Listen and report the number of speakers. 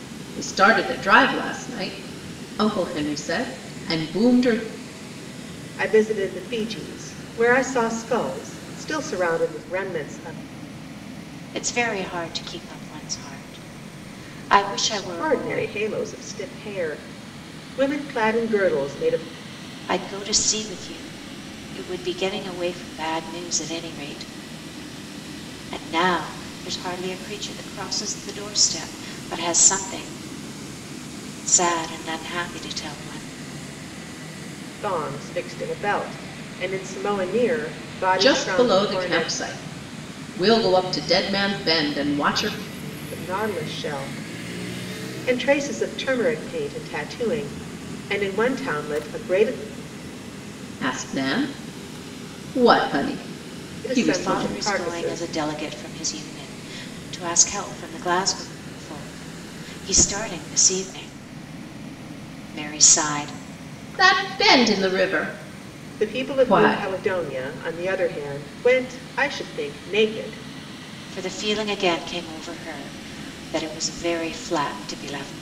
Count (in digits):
3